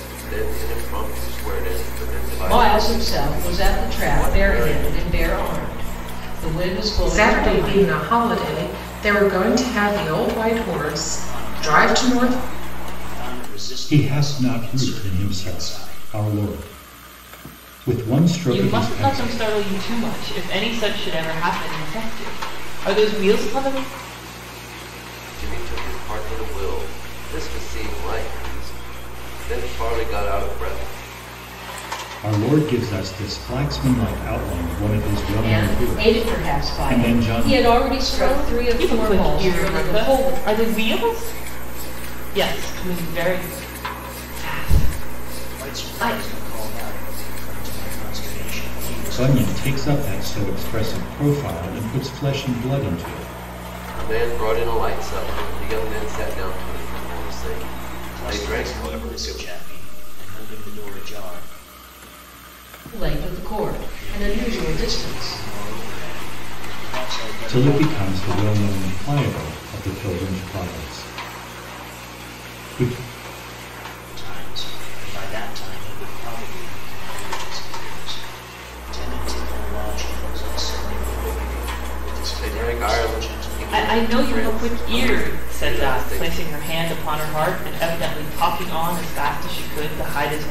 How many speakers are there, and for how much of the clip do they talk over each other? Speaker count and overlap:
6, about 29%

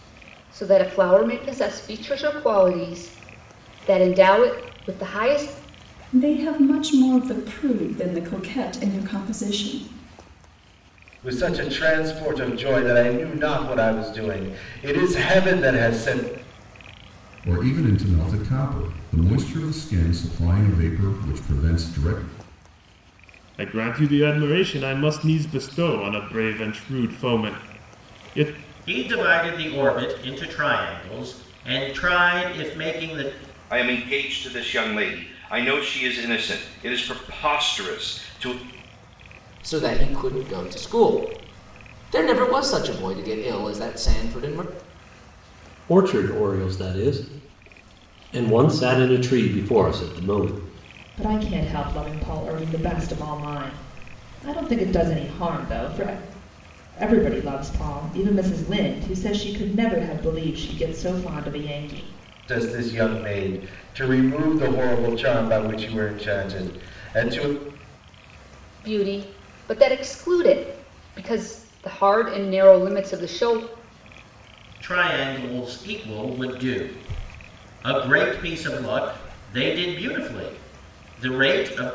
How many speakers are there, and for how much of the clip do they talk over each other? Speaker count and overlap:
10, no overlap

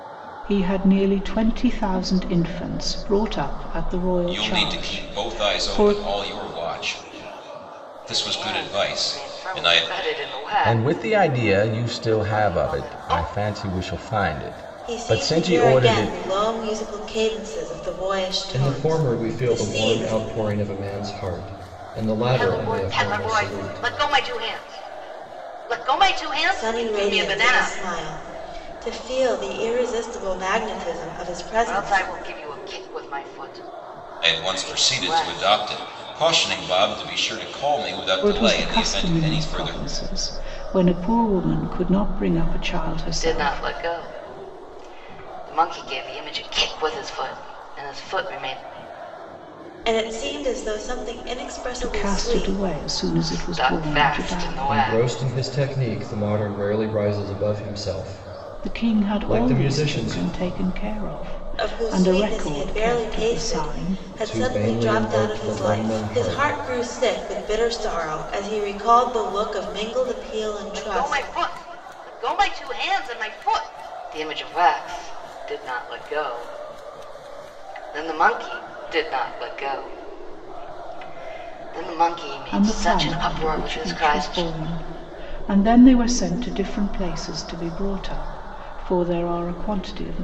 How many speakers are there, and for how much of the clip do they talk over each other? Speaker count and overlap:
6, about 31%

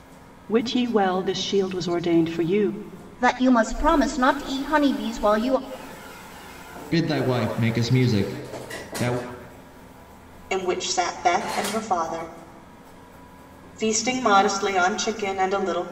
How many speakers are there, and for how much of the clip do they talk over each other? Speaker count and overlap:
4, no overlap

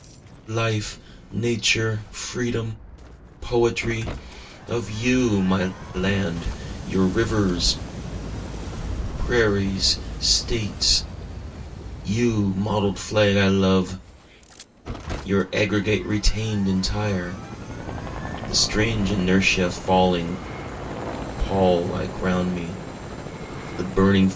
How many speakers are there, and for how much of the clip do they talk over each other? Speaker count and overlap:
1, no overlap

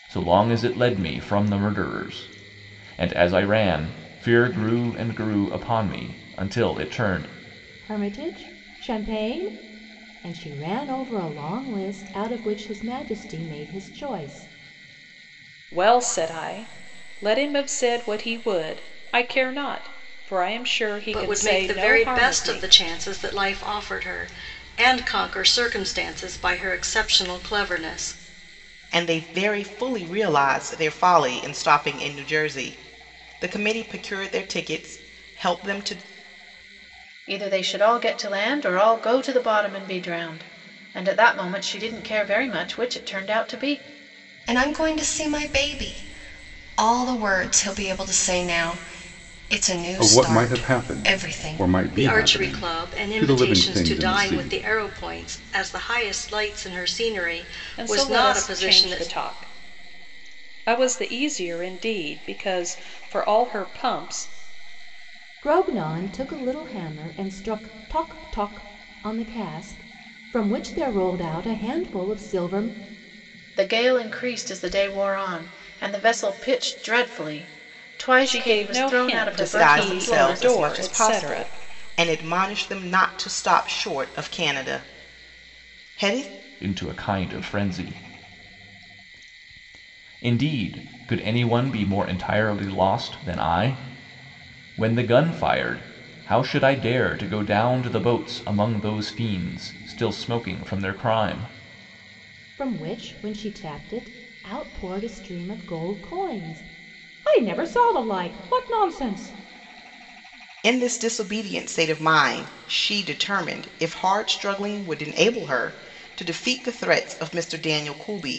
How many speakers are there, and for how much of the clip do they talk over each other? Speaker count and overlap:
8, about 9%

